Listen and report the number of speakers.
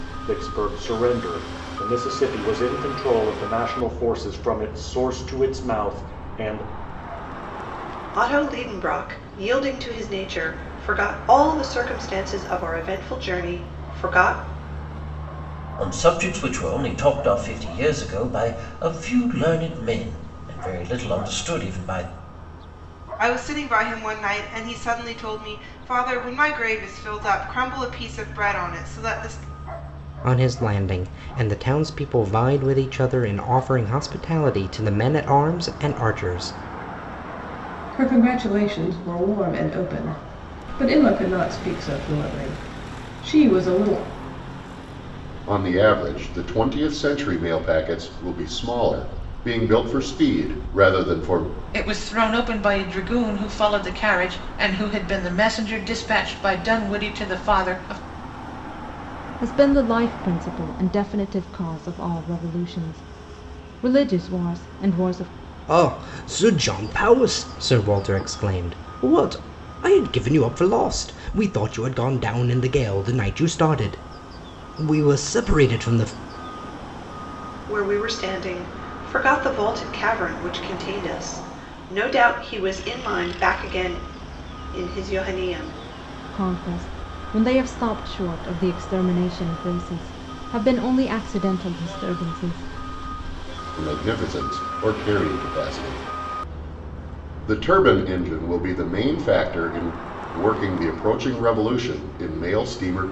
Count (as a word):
nine